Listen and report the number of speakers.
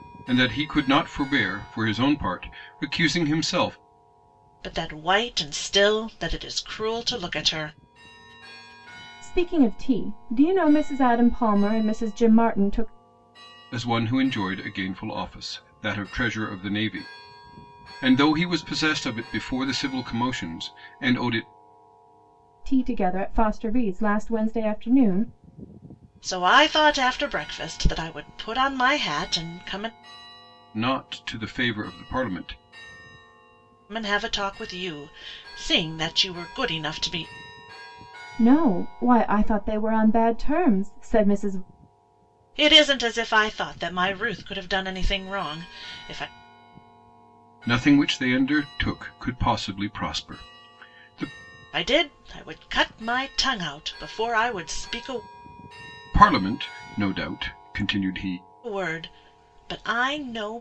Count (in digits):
3